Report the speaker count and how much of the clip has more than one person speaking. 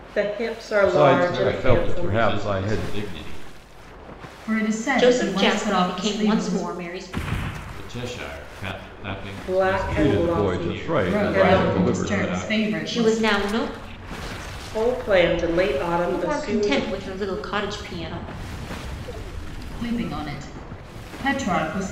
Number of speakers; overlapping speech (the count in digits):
5, about 39%